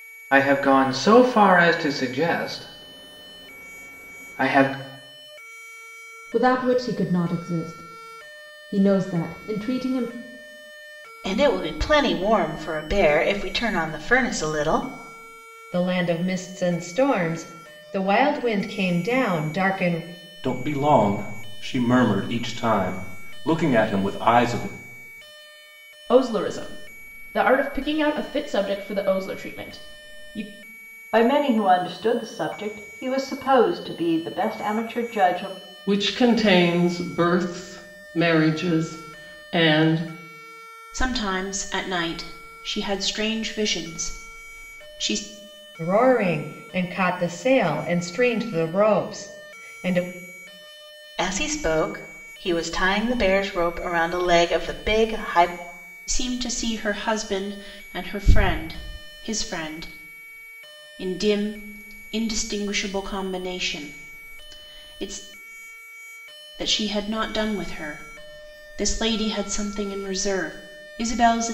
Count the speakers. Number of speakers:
nine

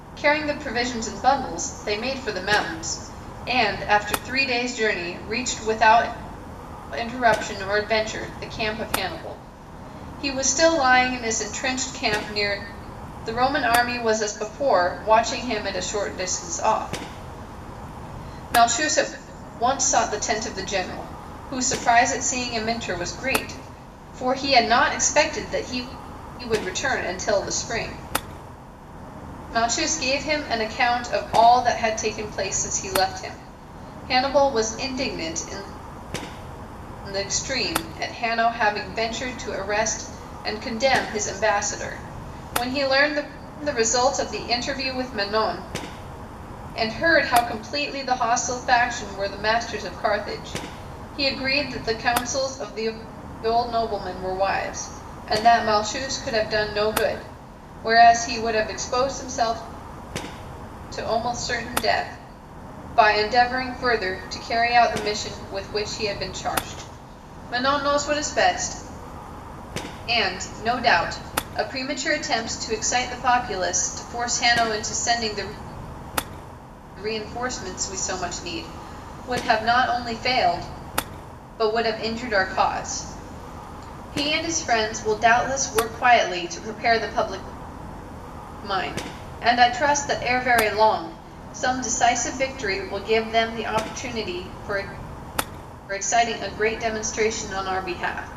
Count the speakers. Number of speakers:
one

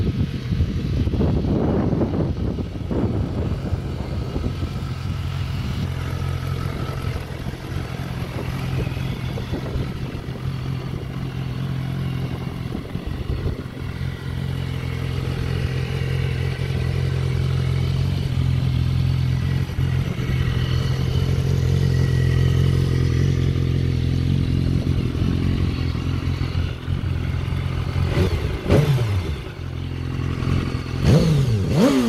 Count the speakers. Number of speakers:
zero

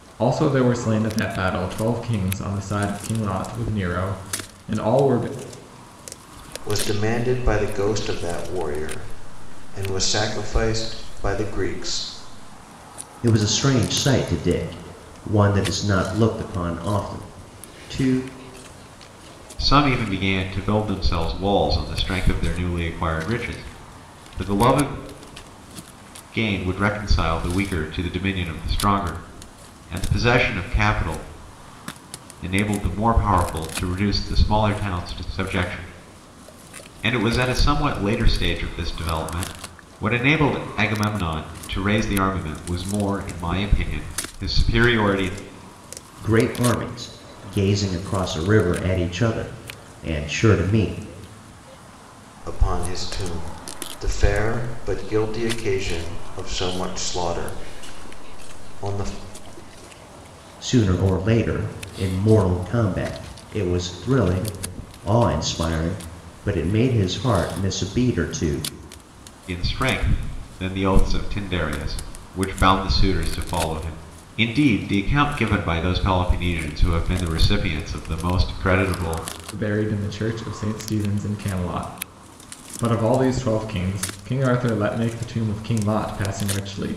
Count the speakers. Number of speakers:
four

